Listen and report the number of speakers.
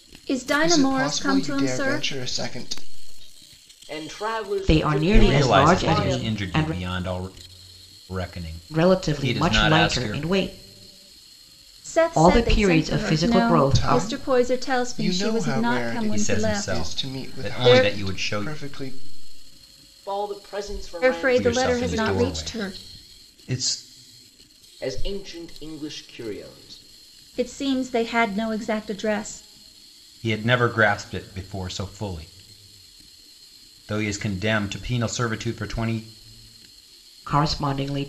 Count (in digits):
5